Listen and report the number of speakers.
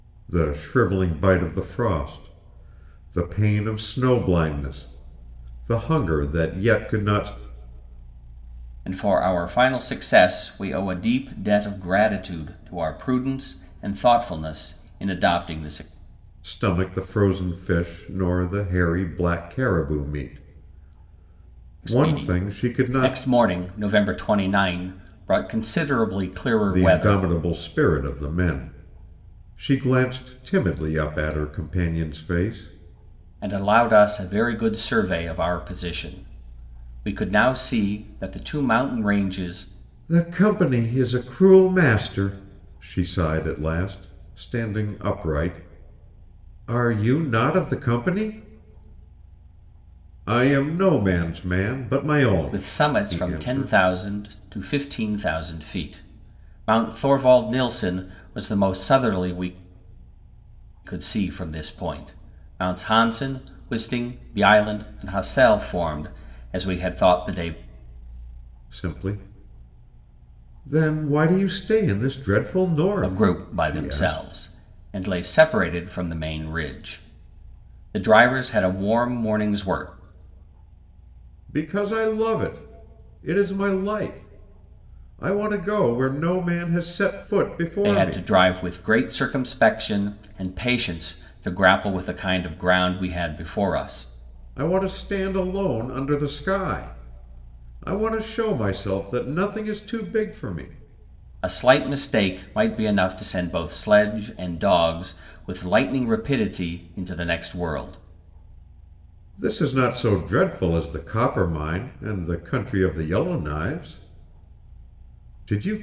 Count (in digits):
2